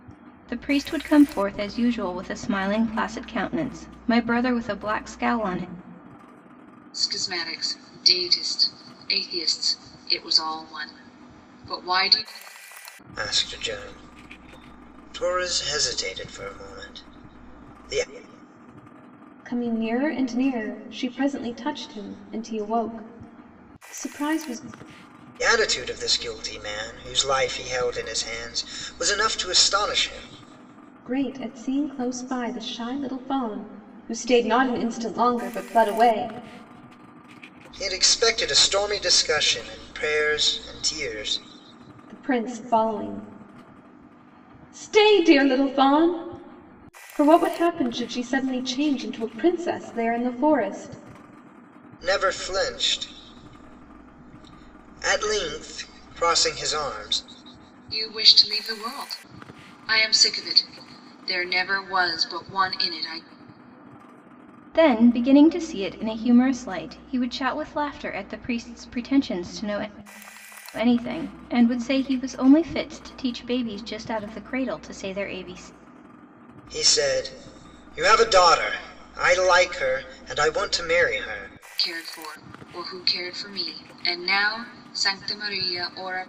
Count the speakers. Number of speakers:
four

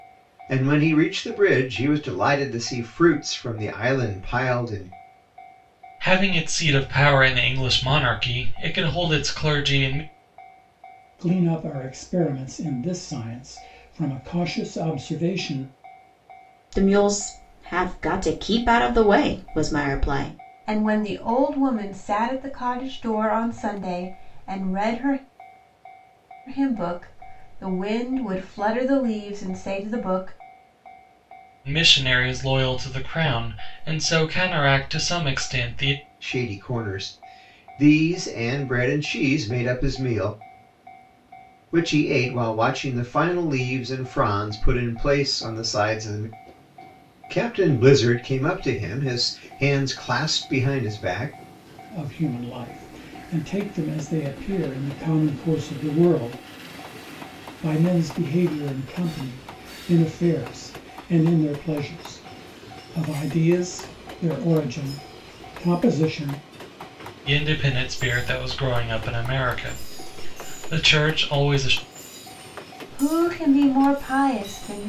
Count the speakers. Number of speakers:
five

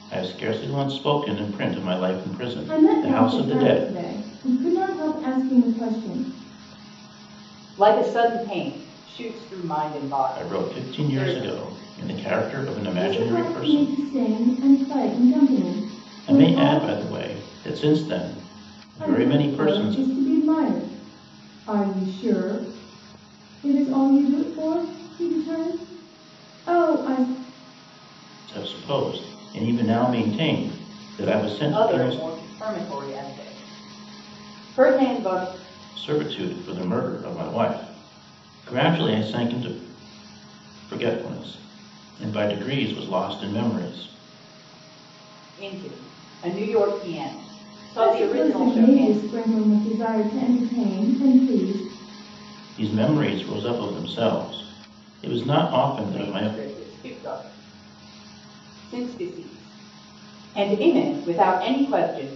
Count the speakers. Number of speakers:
three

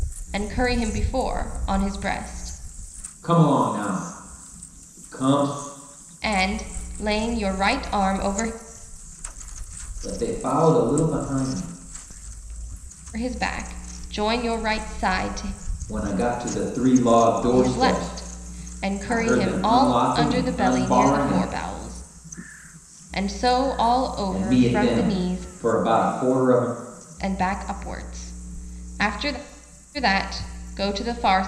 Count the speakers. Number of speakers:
two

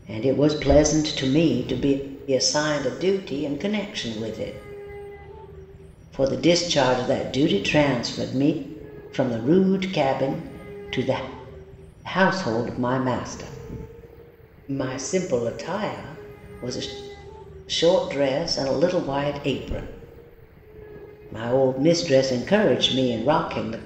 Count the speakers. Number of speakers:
one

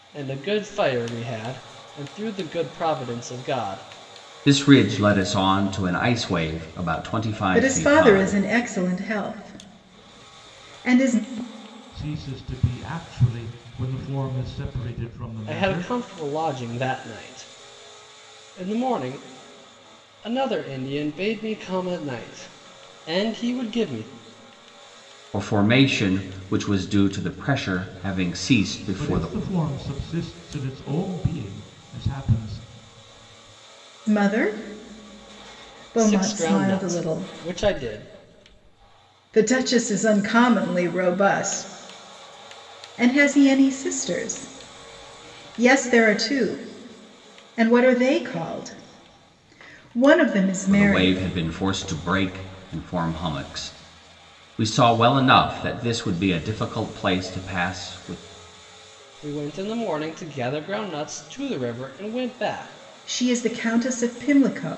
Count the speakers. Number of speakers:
four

